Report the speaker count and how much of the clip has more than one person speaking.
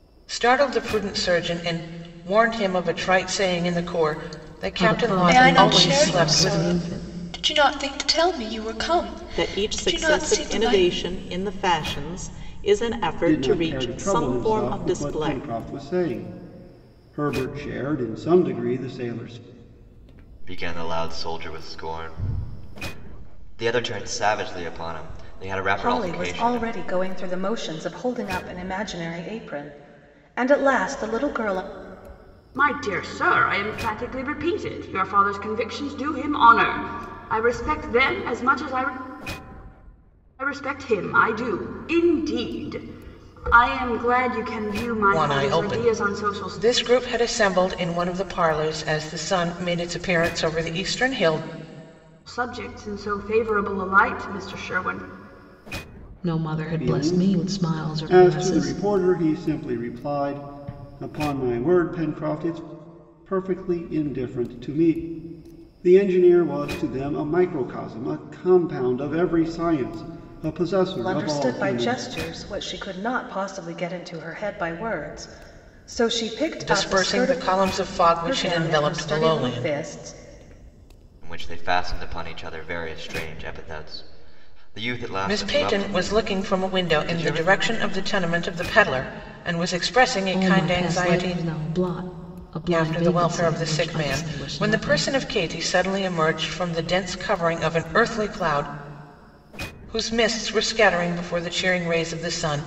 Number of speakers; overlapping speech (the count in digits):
8, about 20%